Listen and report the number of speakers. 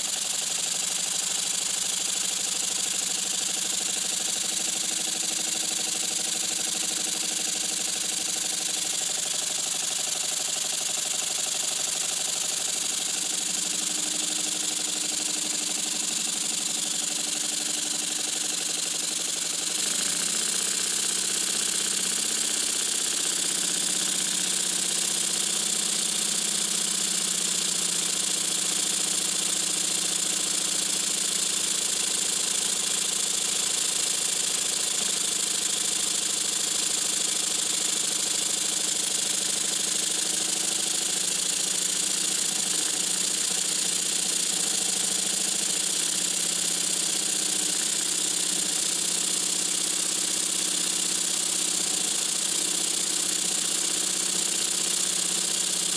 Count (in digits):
0